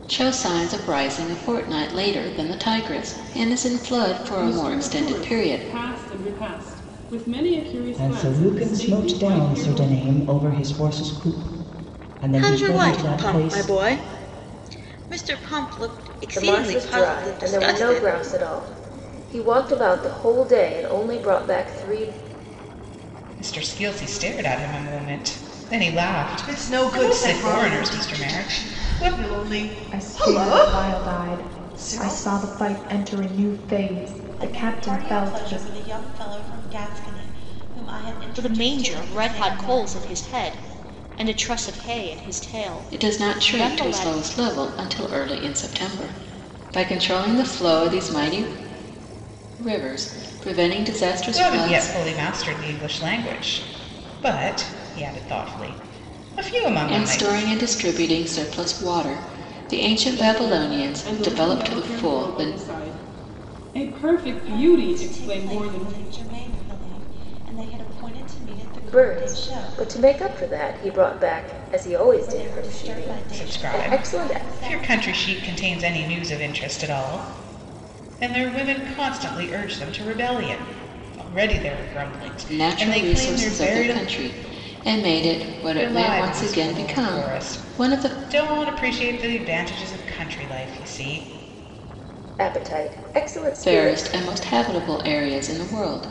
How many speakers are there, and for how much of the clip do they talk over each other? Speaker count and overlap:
ten, about 31%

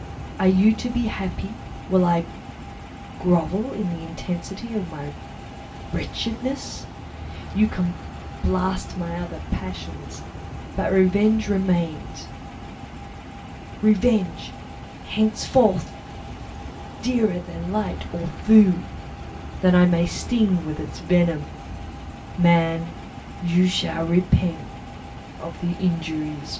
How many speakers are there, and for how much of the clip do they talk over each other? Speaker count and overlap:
one, no overlap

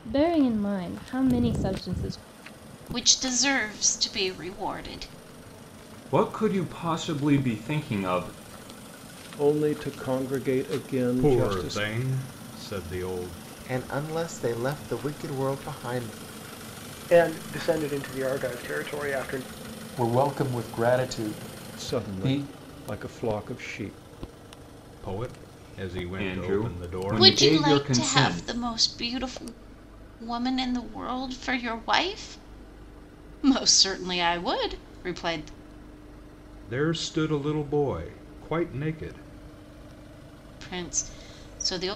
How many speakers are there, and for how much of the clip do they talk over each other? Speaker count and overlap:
eight, about 9%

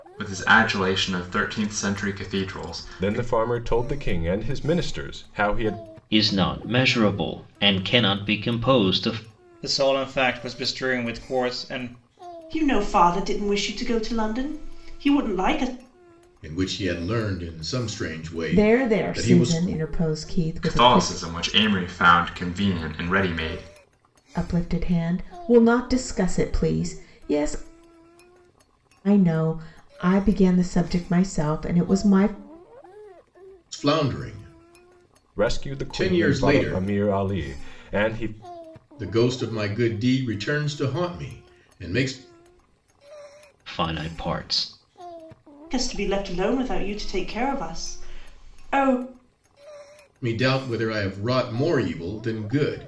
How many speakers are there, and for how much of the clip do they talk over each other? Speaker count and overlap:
seven, about 7%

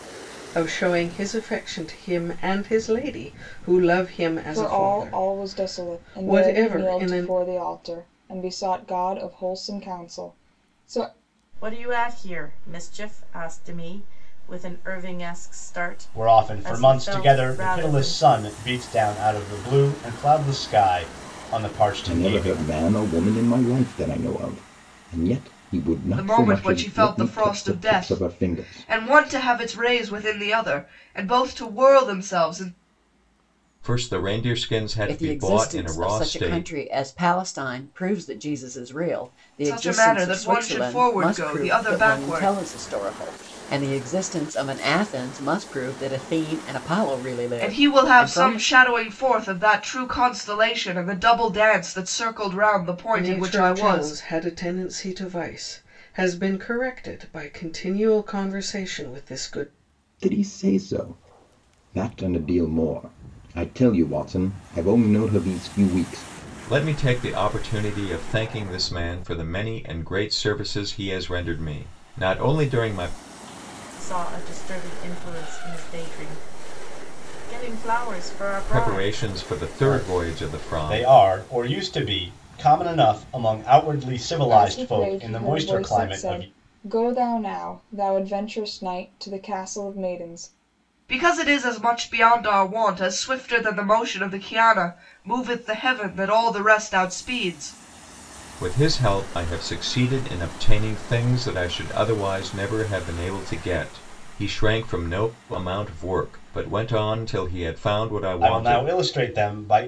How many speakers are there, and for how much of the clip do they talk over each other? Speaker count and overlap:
eight, about 18%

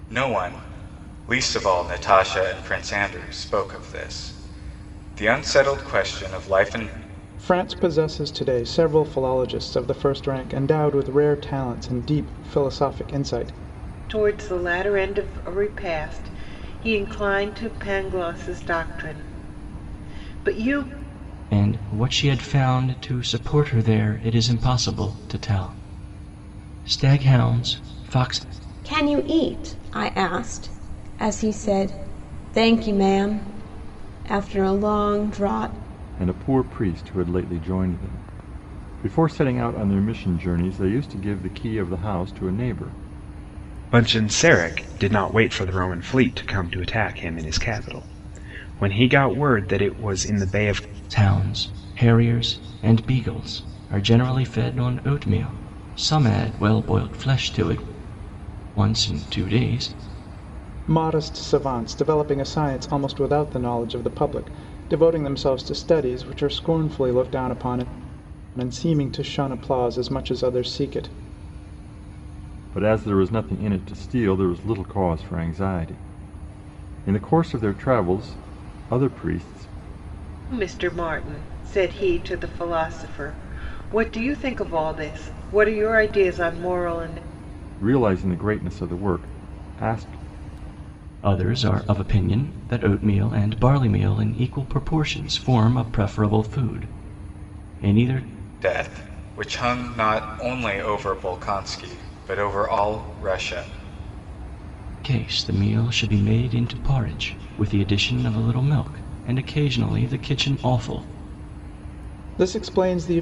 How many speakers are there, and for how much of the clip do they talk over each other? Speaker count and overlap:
seven, no overlap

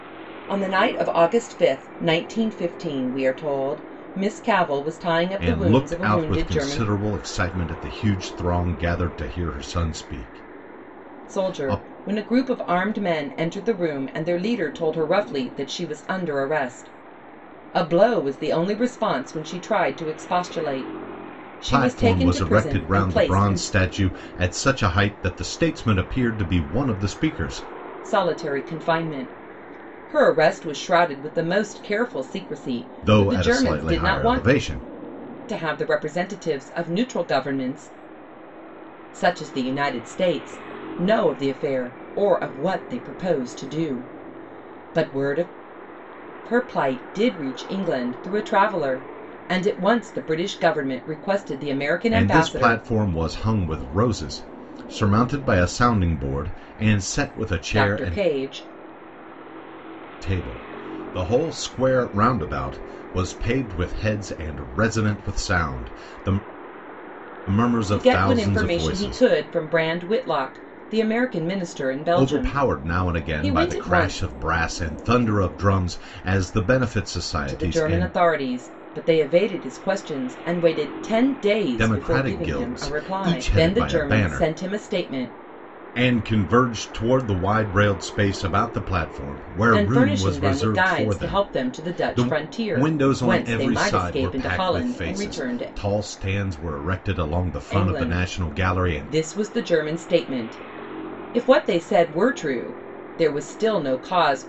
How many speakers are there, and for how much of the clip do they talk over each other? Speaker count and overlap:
two, about 20%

